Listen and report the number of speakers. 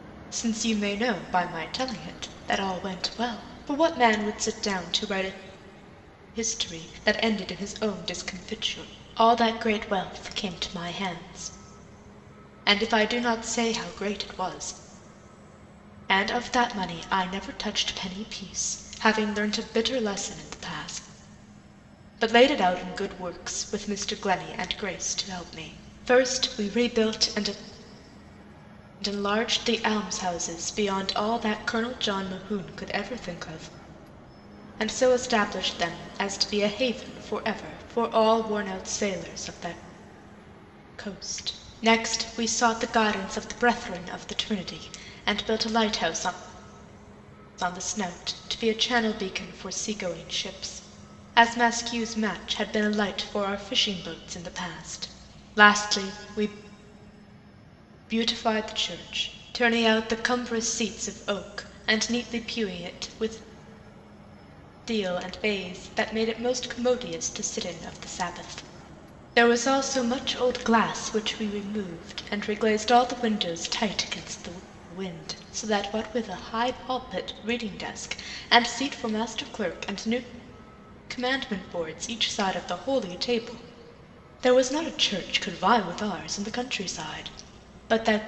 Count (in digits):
1